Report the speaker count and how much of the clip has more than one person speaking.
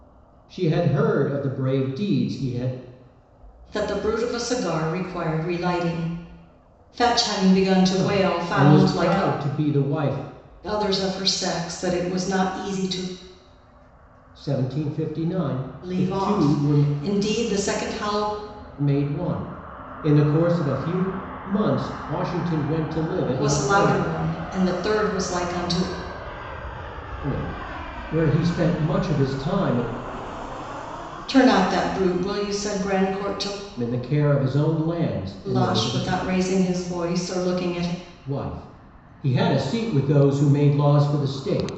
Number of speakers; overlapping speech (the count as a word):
two, about 9%